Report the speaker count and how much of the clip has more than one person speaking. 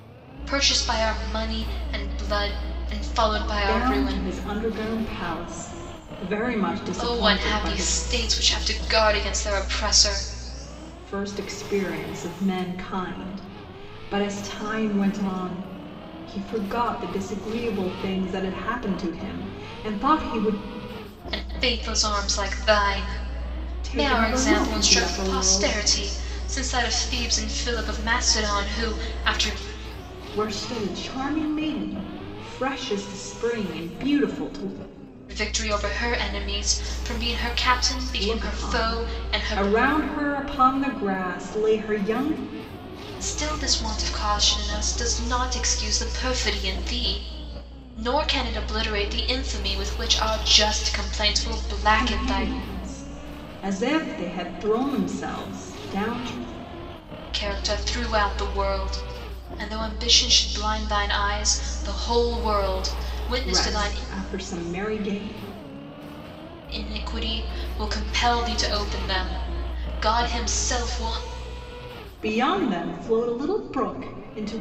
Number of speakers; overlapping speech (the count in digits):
2, about 9%